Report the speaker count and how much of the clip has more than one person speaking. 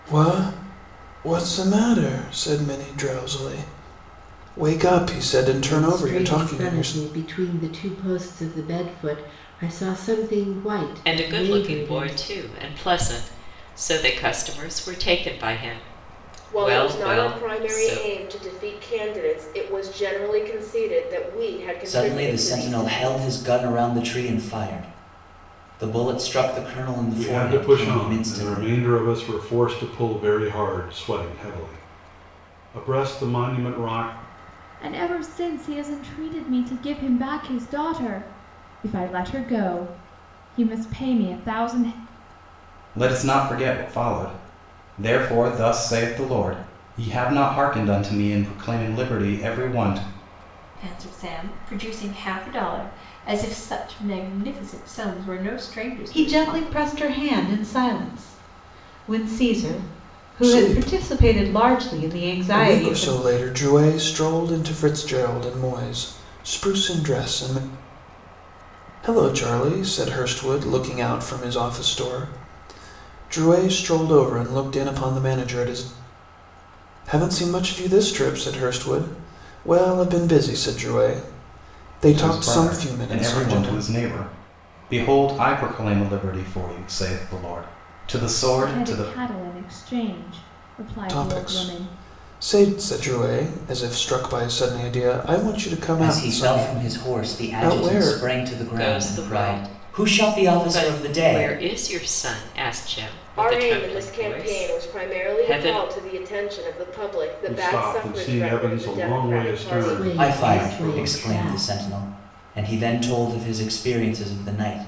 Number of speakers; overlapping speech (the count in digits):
10, about 23%